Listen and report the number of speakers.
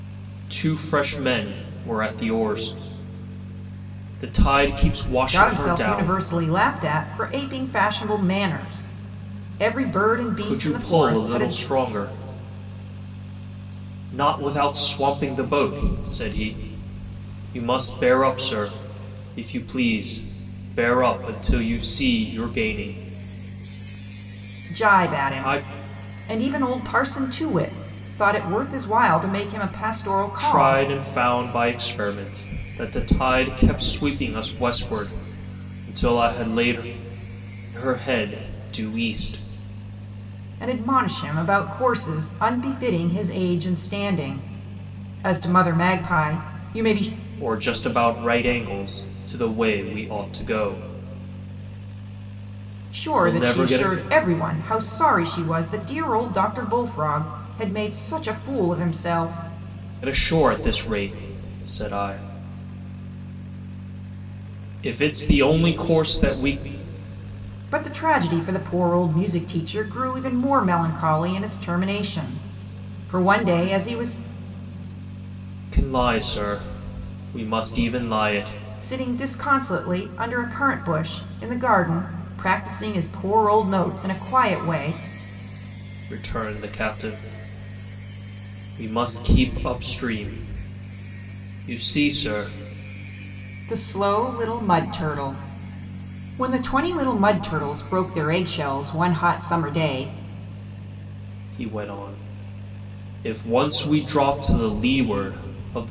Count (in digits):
2